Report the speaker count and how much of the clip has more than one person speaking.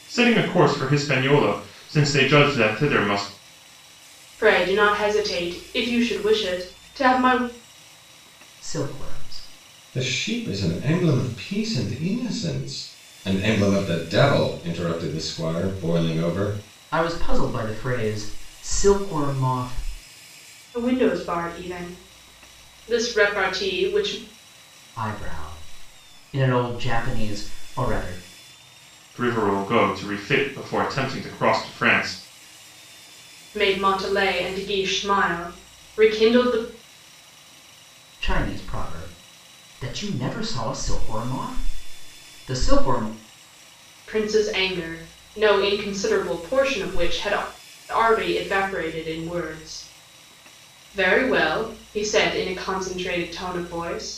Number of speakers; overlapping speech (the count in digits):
4, no overlap